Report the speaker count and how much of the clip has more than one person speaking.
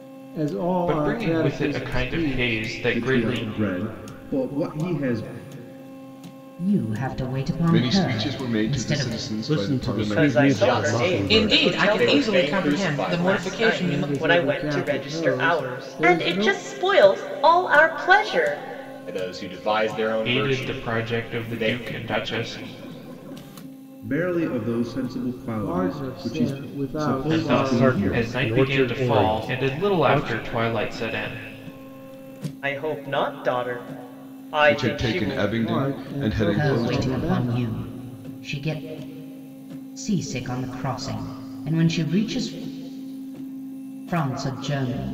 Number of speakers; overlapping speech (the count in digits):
9, about 45%